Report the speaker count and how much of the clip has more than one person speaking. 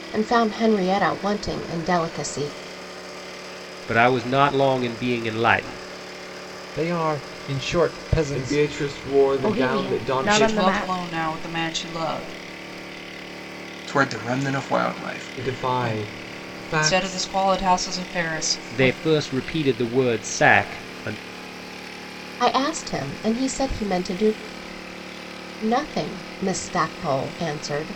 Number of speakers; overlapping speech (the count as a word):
seven, about 13%